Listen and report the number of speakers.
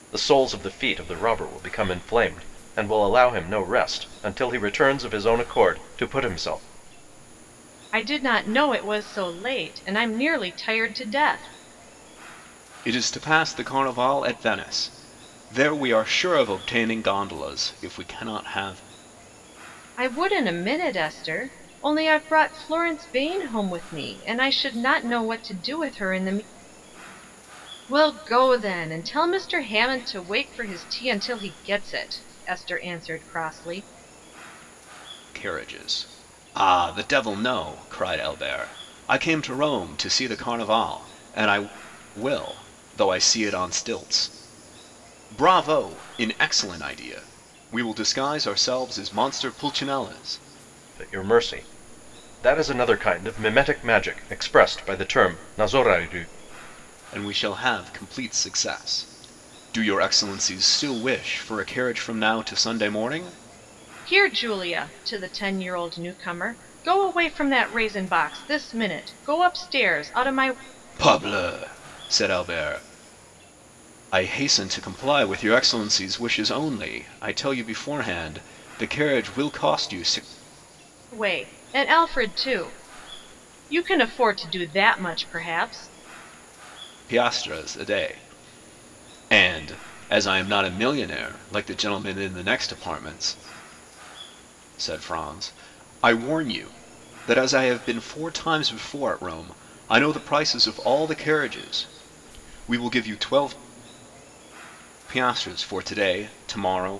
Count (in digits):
3